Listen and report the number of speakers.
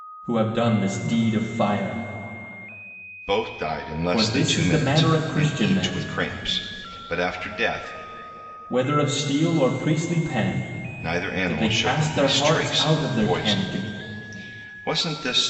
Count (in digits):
2